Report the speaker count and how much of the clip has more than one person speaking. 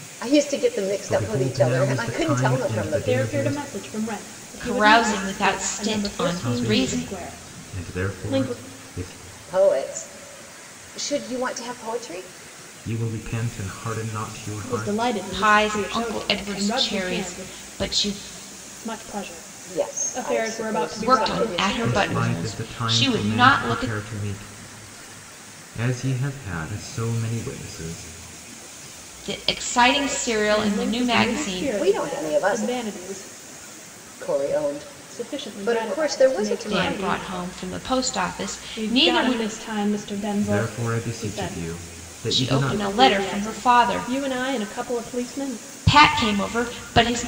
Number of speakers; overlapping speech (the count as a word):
four, about 48%